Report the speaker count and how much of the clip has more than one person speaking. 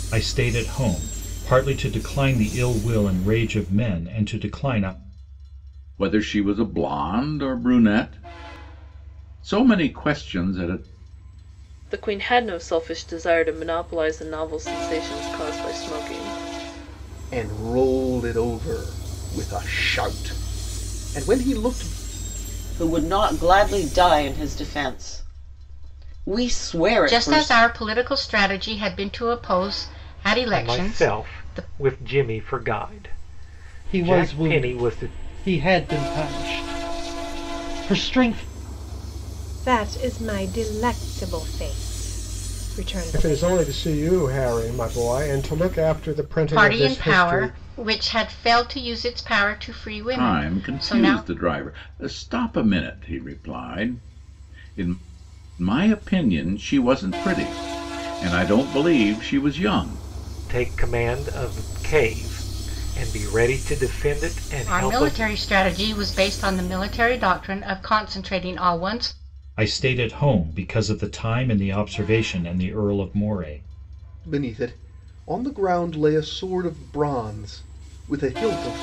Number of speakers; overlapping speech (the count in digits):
10, about 8%